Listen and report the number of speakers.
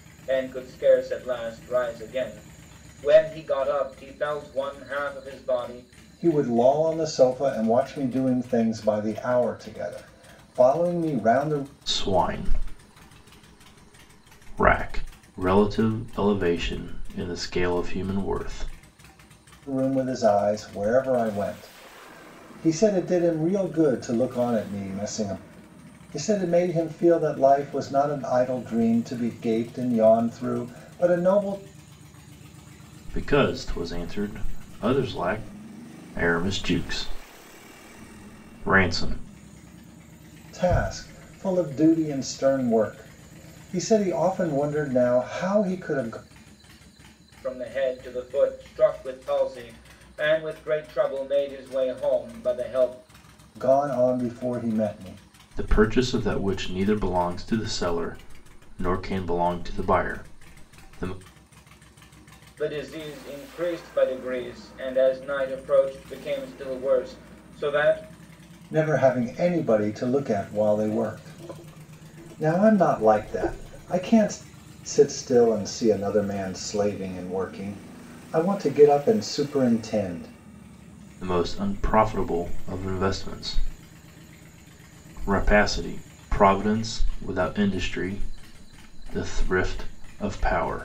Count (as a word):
three